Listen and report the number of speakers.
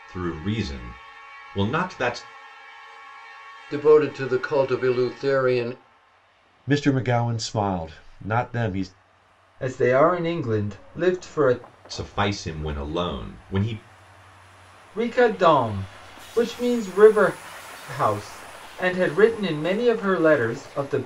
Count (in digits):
4